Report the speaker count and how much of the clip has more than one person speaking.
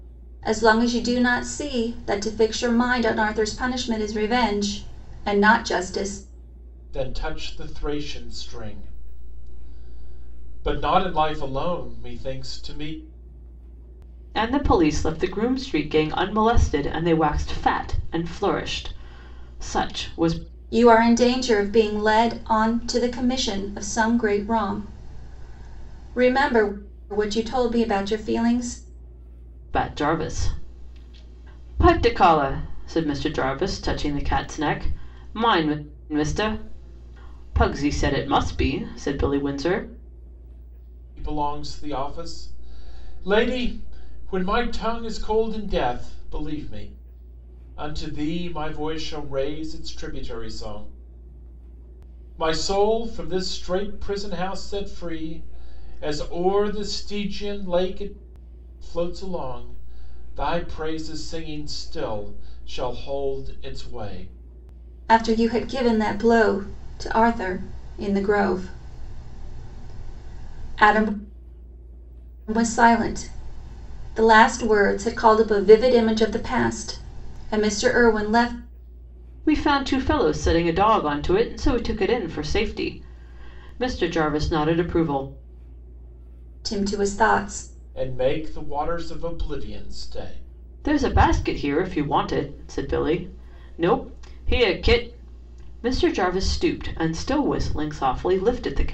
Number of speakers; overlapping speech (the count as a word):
three, no overlap